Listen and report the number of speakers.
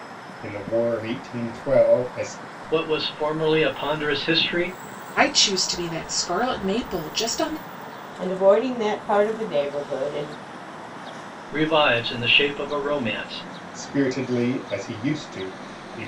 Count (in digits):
4